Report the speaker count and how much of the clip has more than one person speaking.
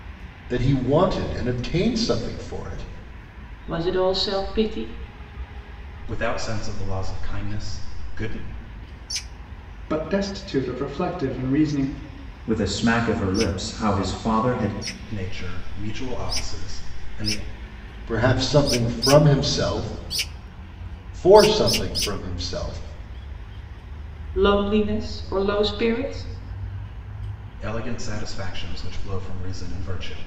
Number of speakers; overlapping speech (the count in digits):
5, no overlap